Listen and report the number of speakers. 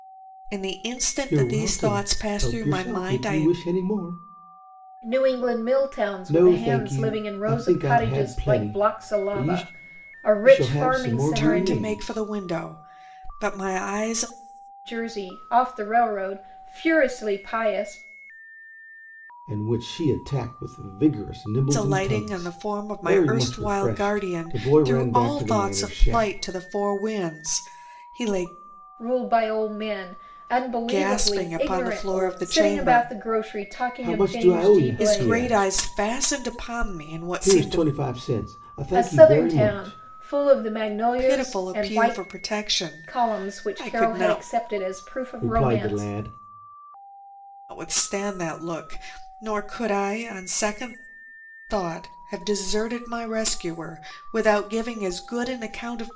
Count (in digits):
3